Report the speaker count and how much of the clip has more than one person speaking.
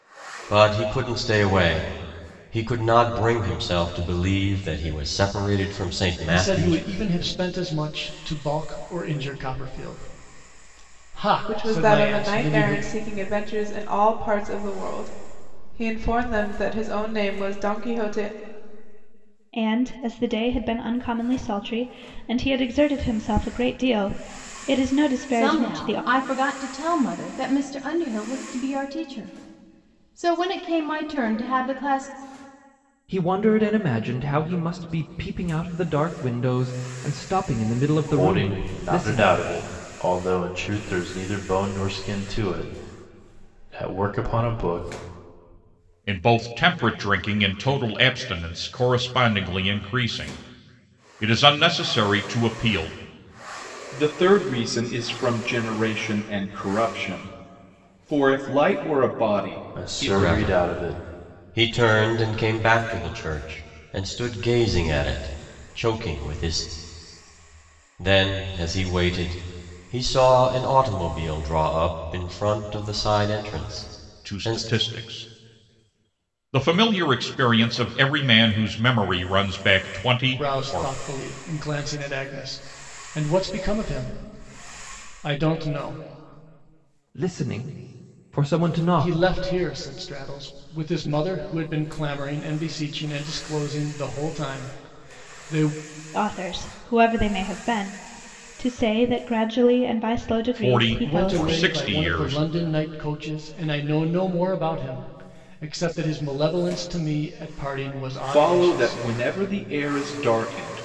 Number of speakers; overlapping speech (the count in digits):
9, about 9%